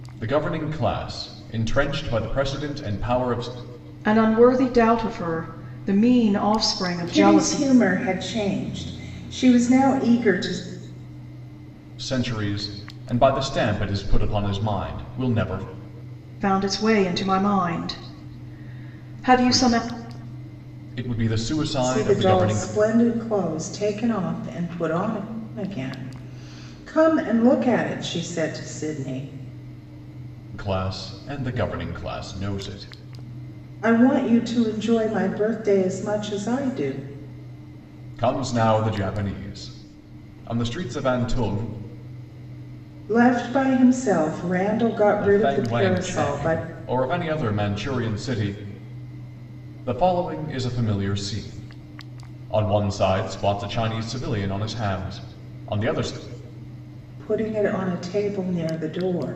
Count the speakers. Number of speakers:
3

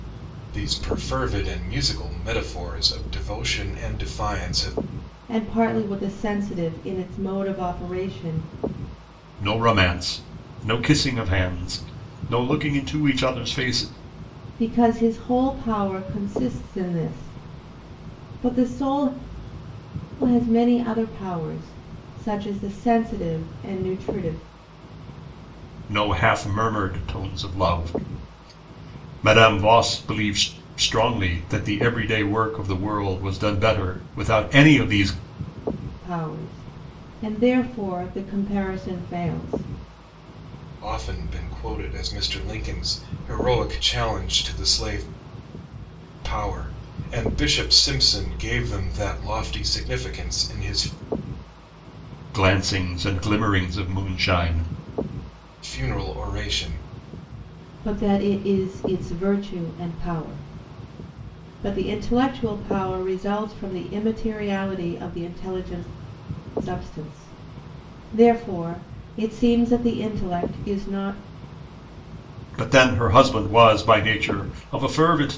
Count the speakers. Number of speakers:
3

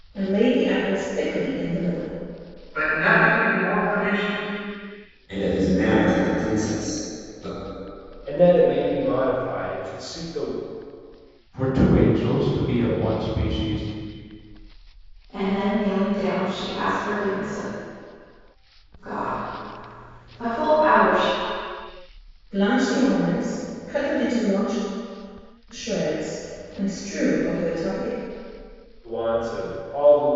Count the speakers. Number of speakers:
6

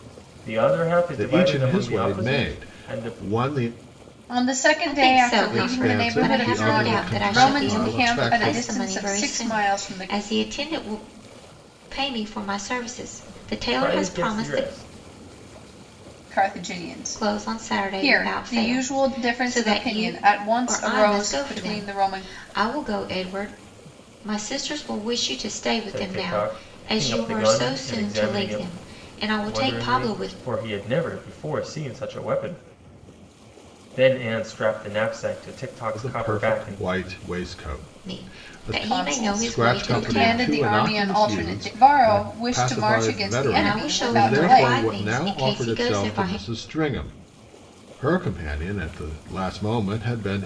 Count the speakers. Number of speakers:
4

